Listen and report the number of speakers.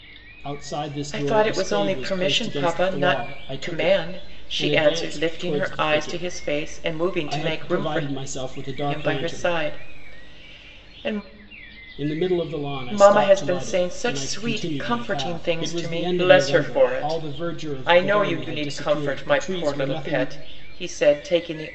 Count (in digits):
2